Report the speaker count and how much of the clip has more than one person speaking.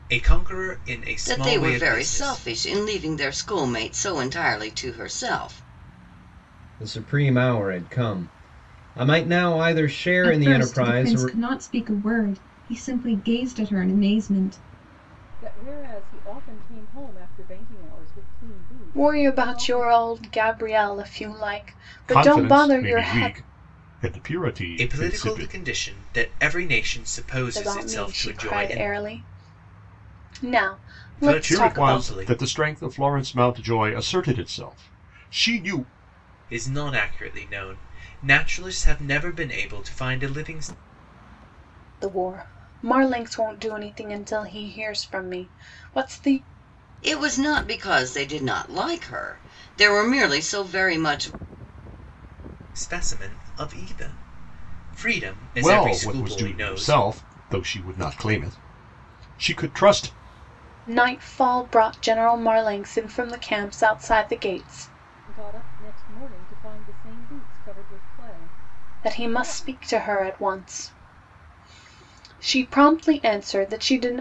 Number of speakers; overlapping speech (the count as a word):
seven, about 14%